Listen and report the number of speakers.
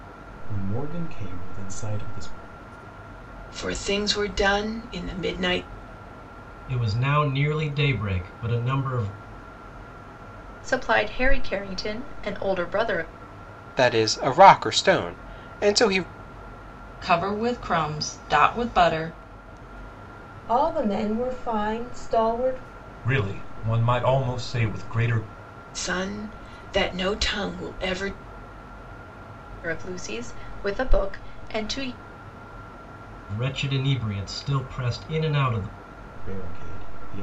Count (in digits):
8